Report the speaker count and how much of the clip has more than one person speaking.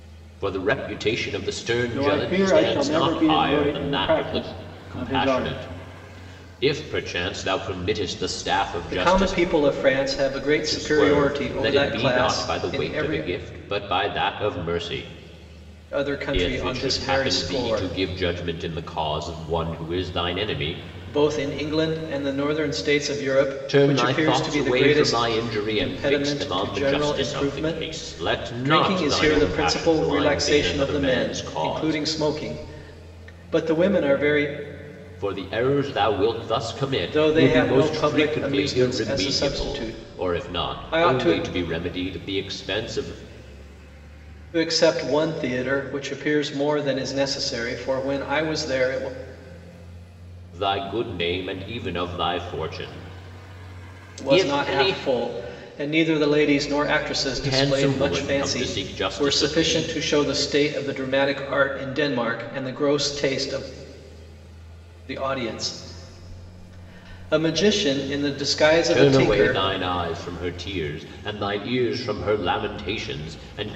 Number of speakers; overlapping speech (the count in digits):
2, about 33%